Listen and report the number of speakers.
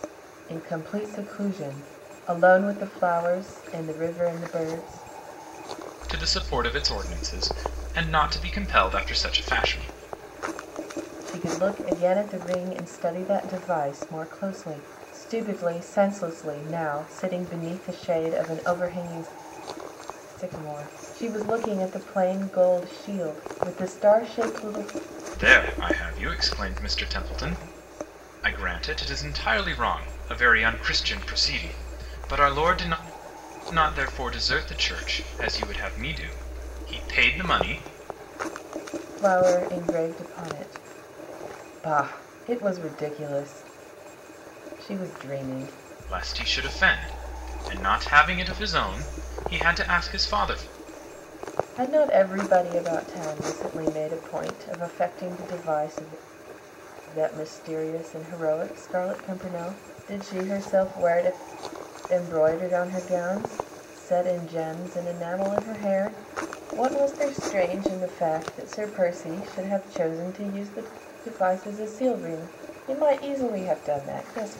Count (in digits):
2